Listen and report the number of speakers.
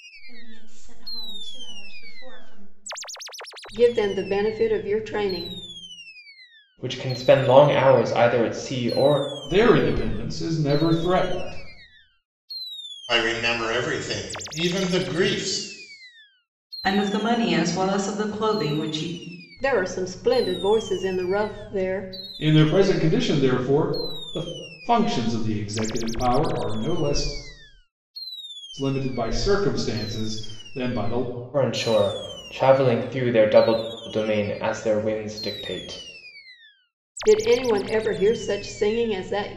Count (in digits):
6